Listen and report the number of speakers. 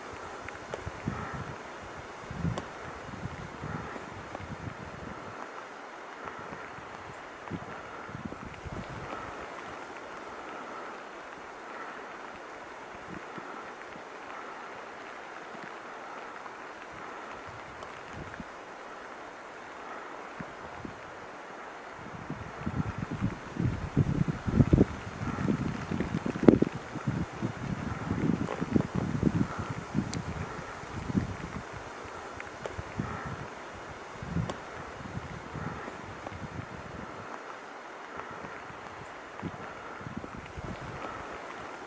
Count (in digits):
0